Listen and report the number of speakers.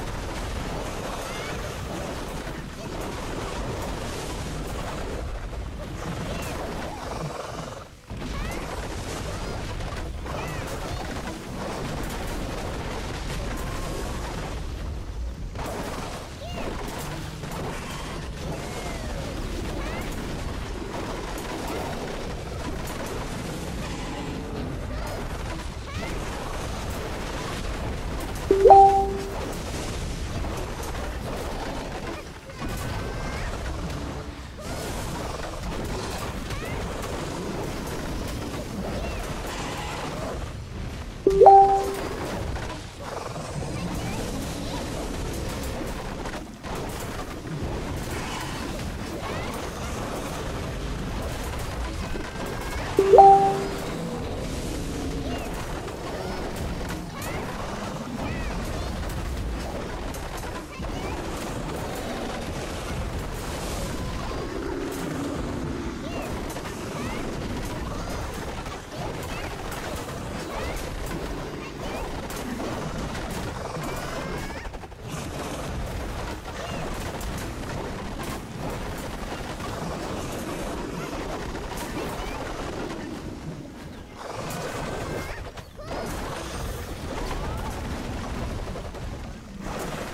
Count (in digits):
0